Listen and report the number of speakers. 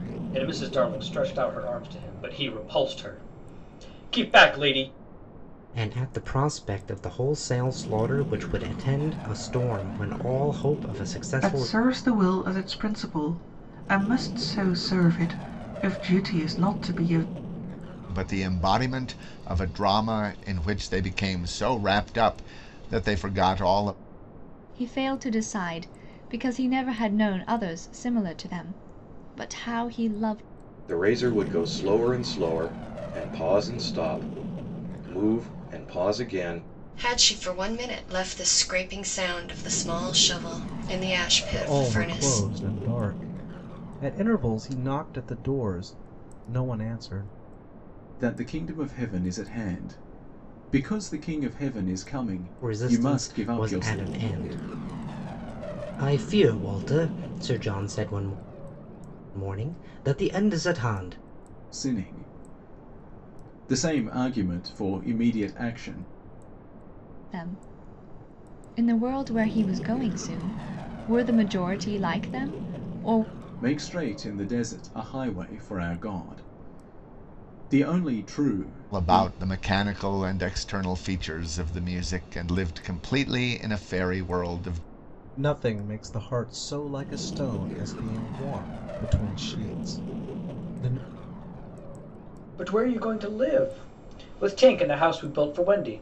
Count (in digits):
9